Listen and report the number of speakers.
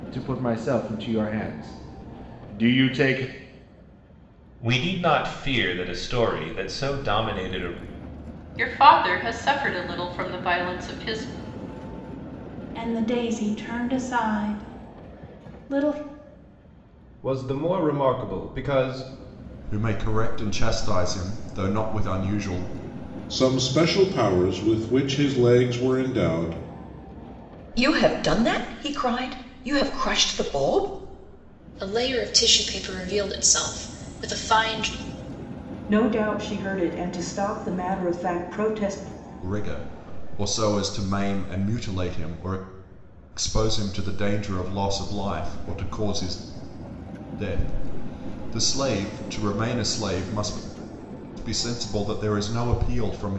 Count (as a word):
ten